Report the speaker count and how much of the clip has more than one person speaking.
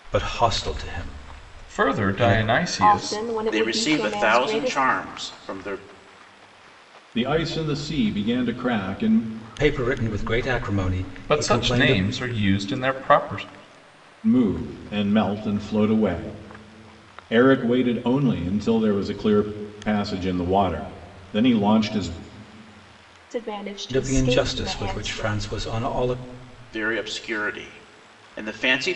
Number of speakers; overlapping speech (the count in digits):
5, about 17%